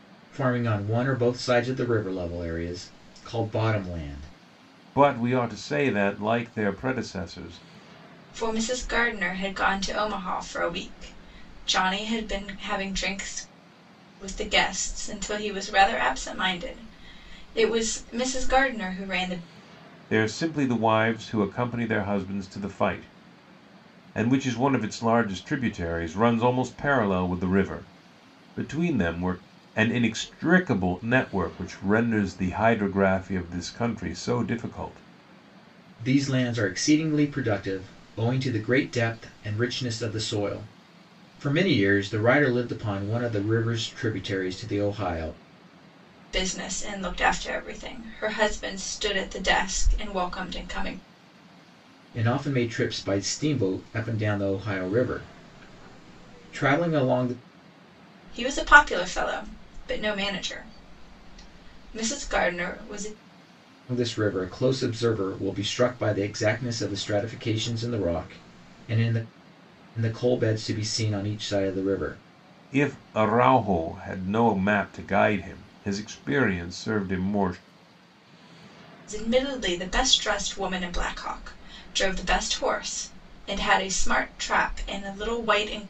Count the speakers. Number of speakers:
3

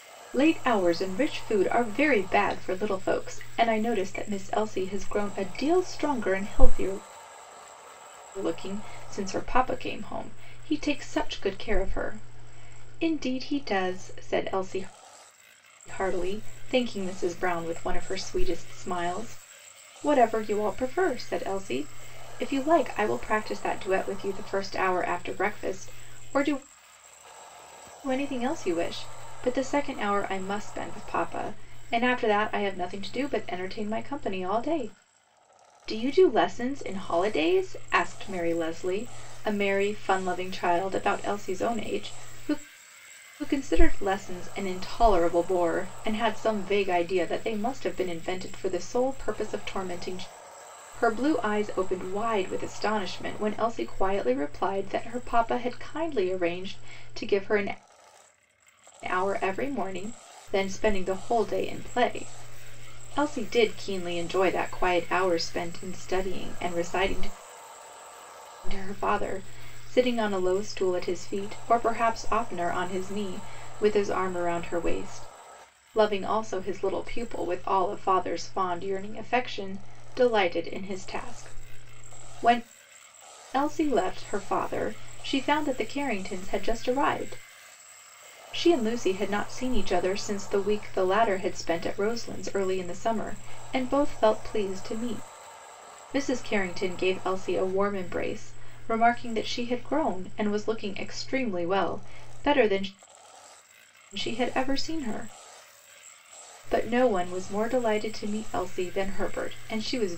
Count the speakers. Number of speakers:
1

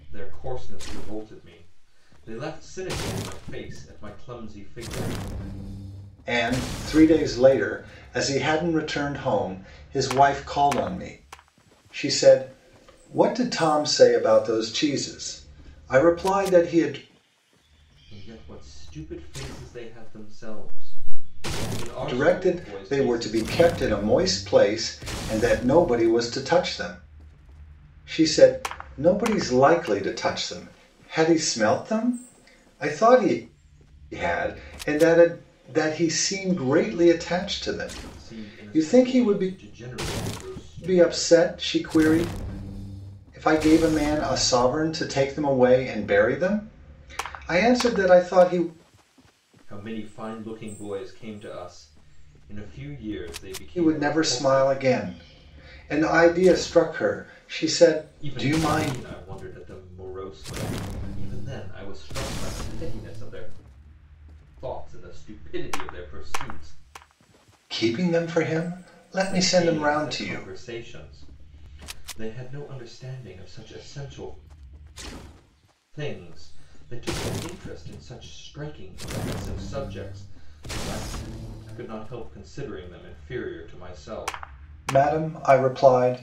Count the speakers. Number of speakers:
2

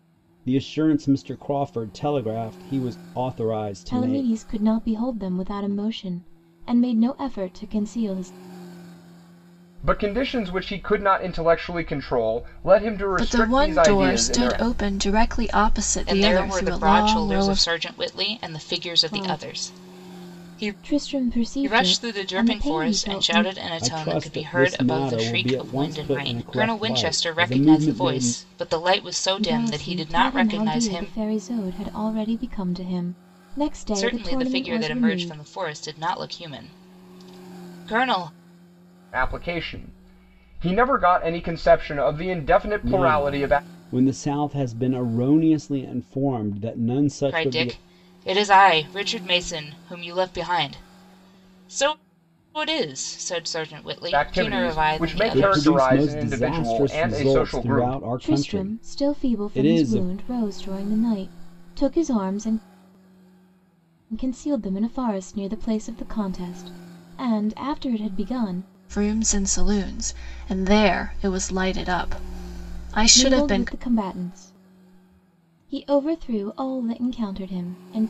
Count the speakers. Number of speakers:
5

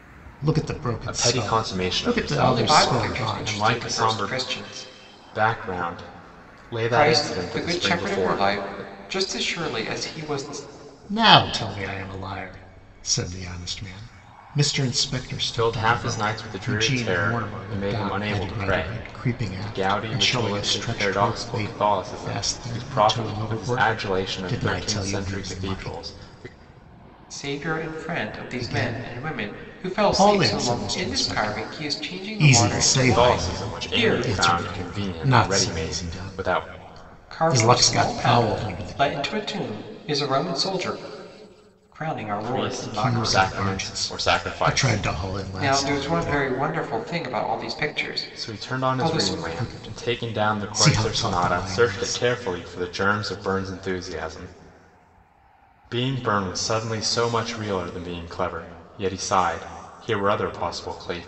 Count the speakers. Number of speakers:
3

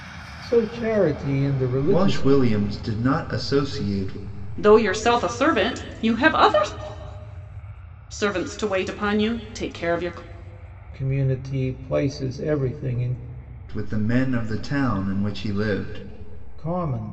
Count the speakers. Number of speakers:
3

